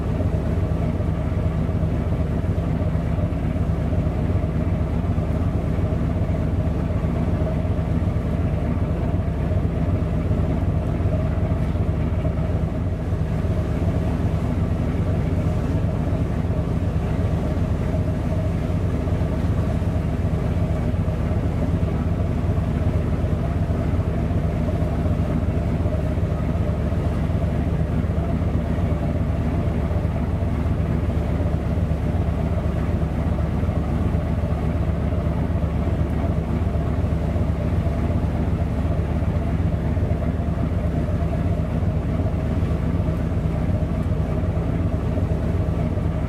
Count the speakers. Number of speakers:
0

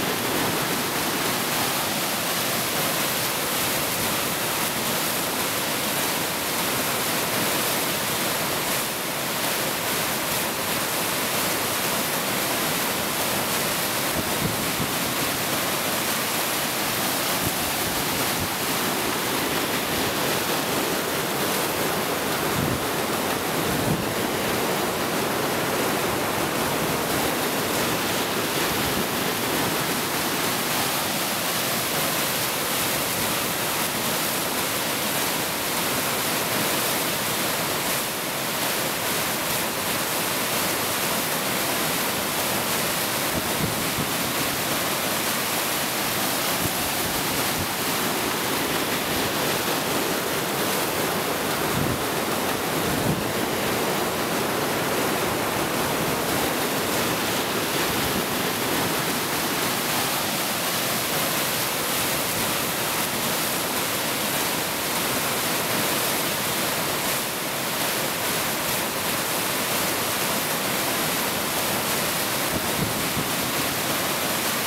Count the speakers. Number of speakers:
0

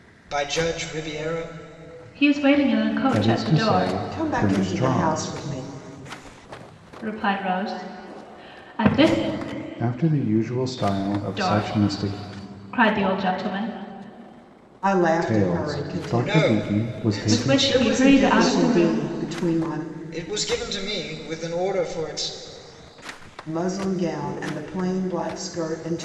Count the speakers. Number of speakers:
4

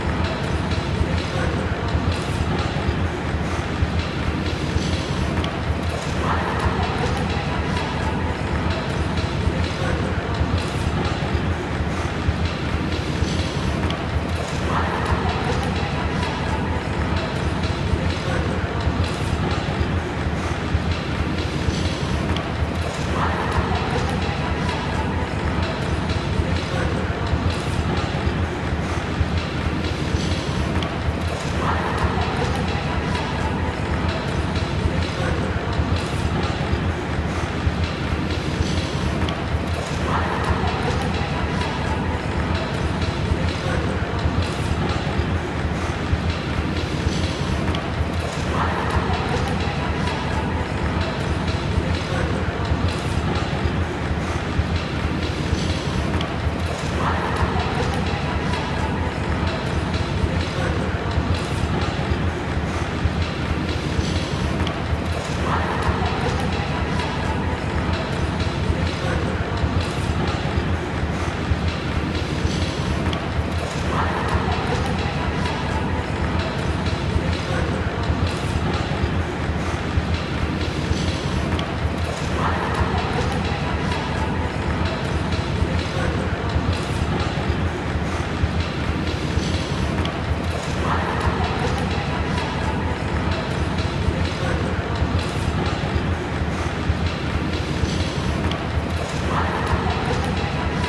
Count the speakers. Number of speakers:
0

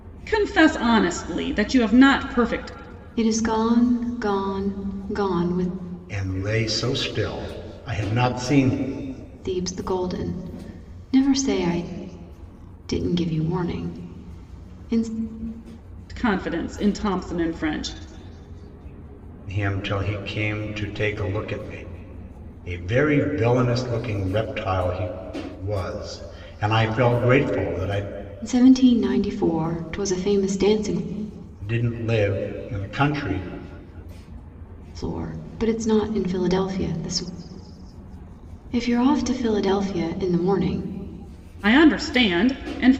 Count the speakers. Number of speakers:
3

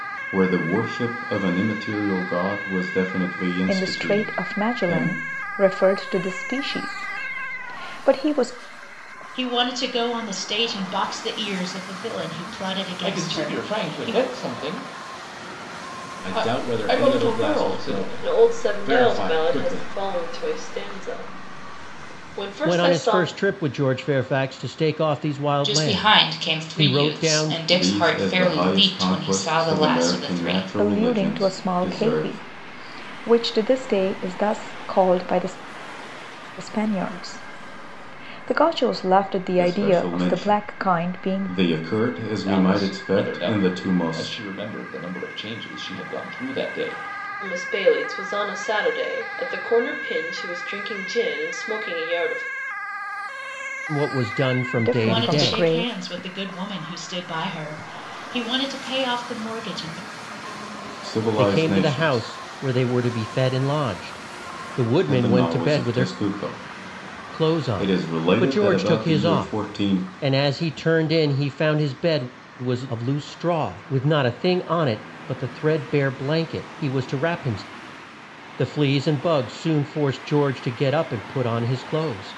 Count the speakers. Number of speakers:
8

